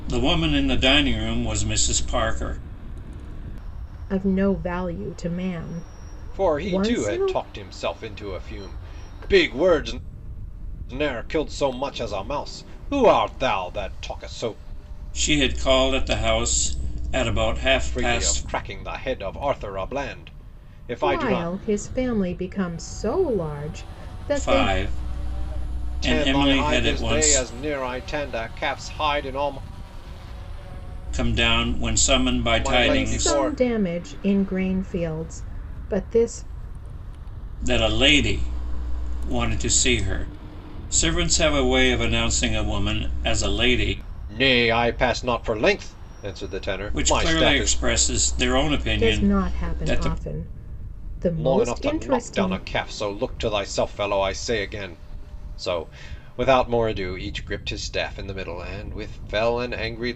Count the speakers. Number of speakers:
three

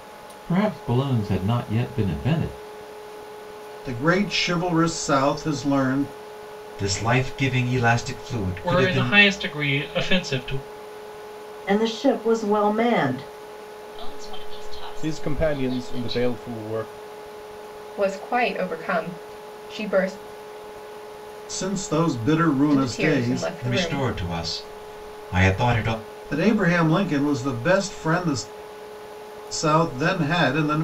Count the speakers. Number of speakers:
eight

